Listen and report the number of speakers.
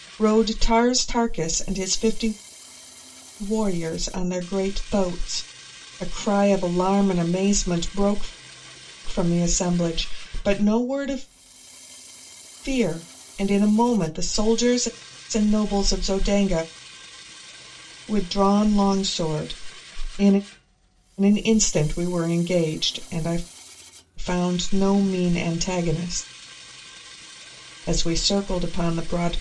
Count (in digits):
1